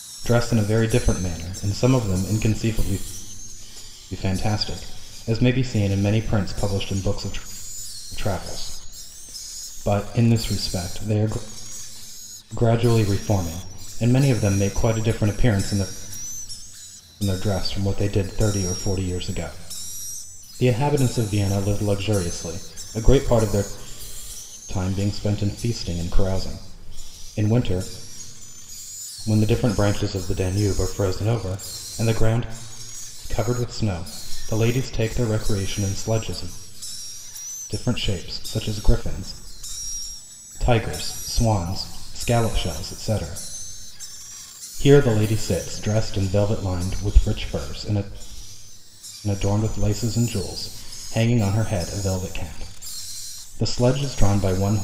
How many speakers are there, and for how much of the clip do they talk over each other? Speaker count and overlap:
1, no overlap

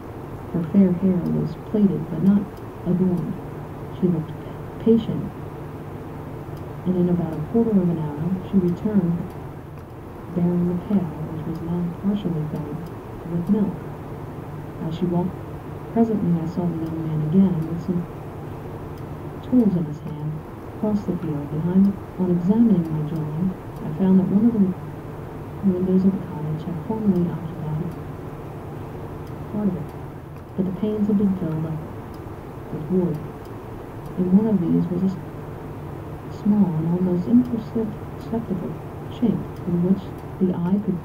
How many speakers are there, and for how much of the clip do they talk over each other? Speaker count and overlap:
1, no overlap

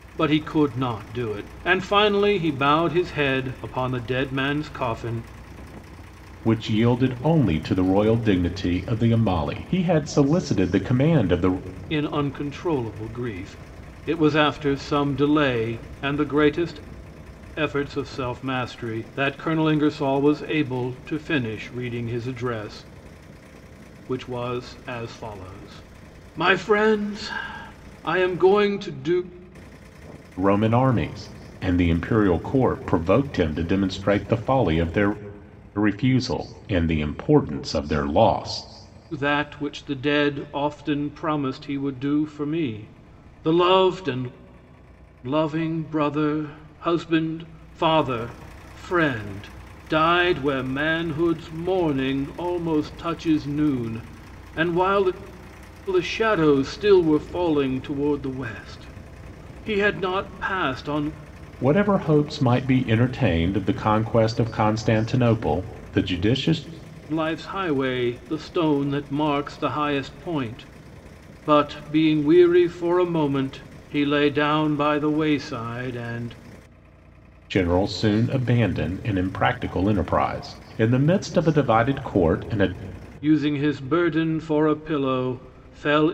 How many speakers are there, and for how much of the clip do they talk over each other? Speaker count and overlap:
2, no overlap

